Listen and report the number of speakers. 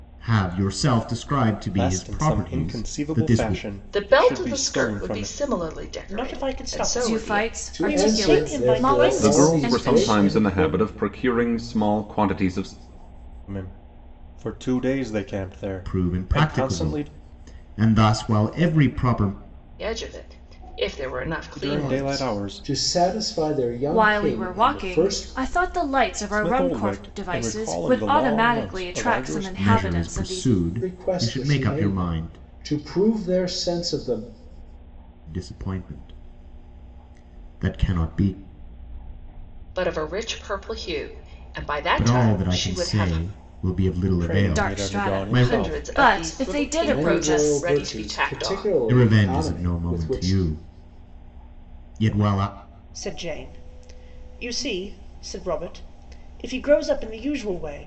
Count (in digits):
7